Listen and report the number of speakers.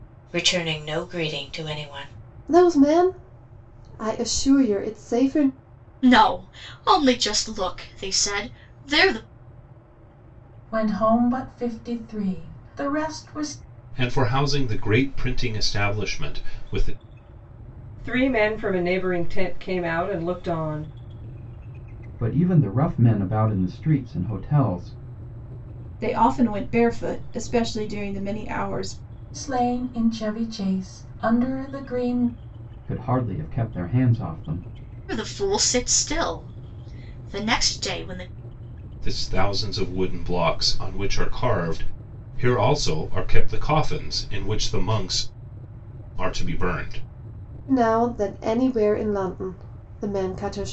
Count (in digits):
8